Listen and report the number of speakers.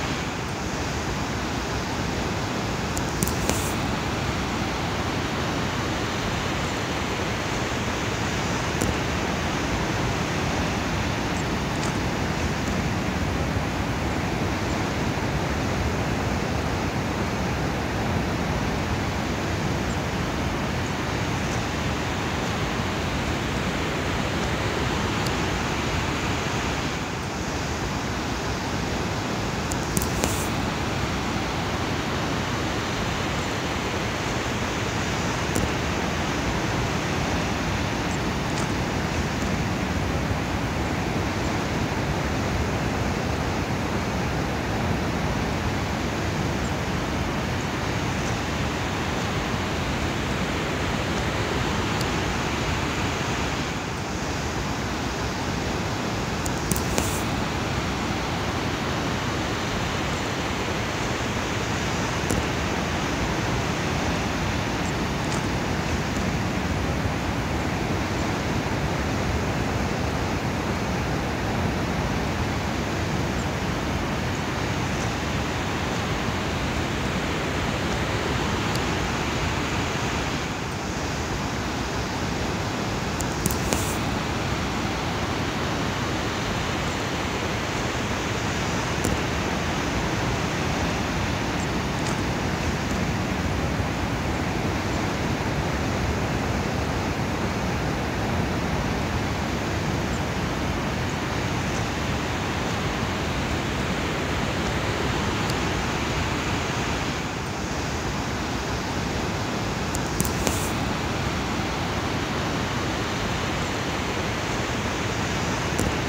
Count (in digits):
0